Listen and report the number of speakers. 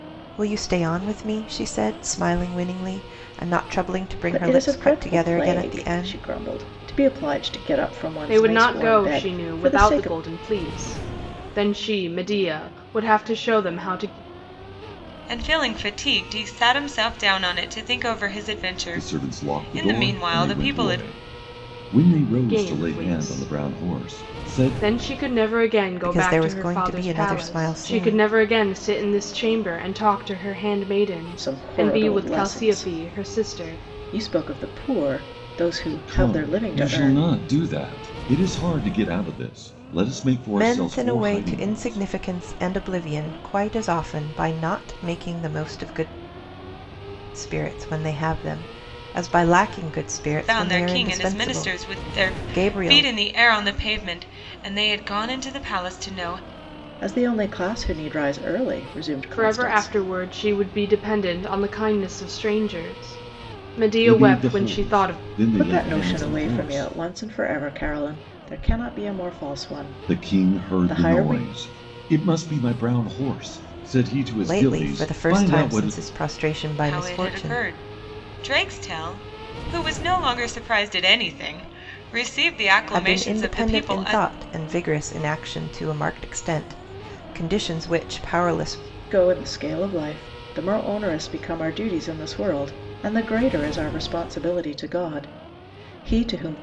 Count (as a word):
five